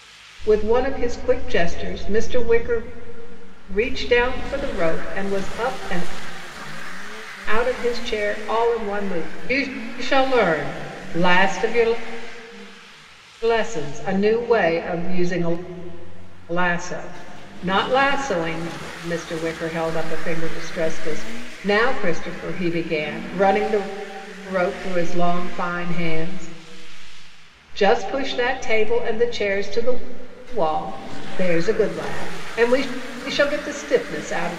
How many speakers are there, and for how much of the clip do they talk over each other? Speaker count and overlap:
1, no overlap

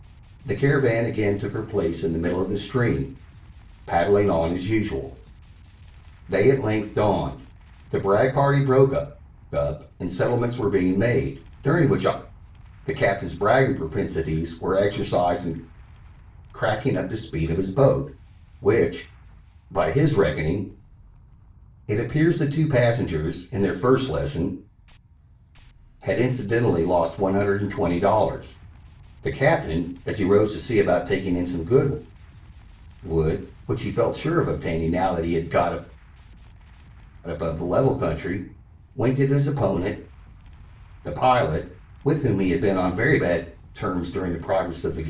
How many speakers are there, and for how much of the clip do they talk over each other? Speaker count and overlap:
1, no overlap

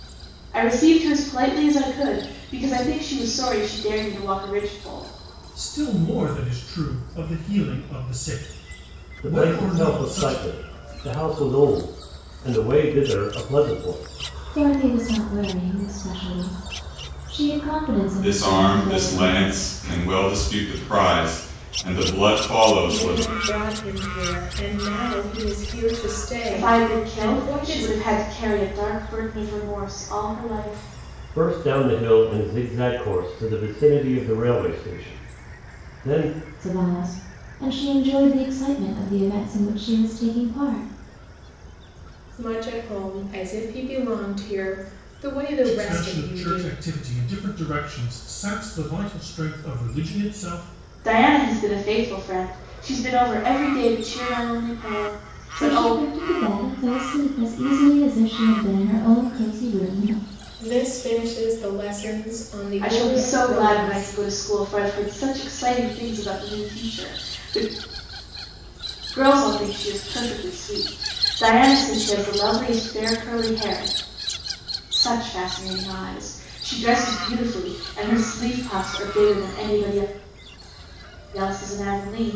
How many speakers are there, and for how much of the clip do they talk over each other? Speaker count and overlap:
6, about 9%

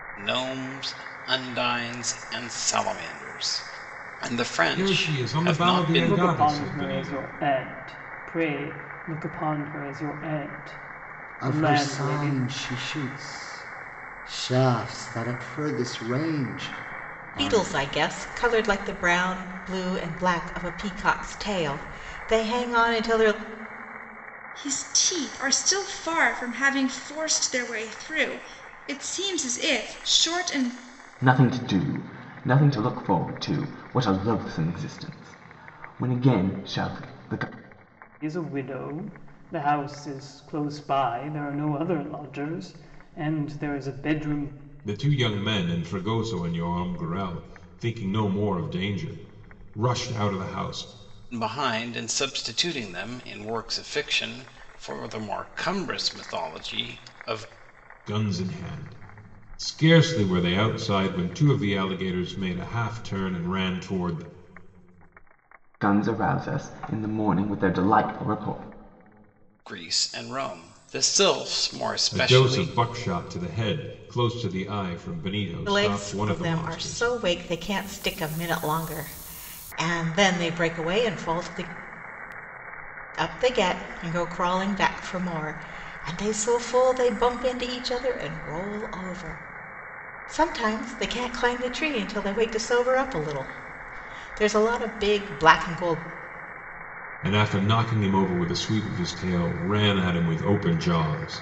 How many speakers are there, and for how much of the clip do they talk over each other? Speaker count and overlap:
7, about 6%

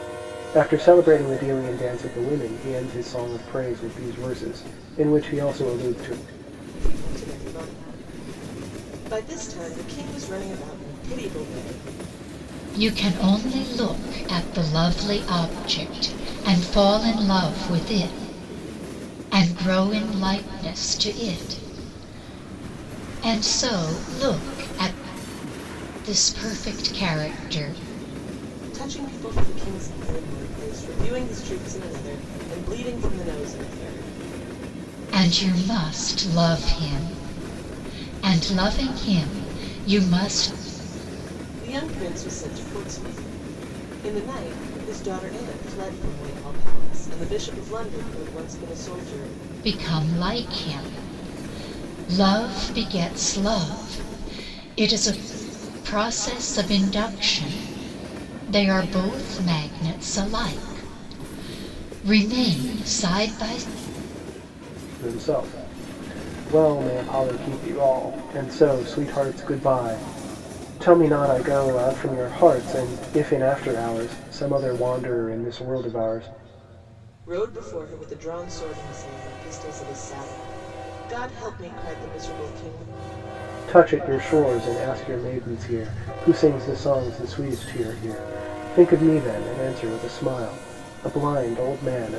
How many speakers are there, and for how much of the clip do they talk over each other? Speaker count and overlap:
3, no overlap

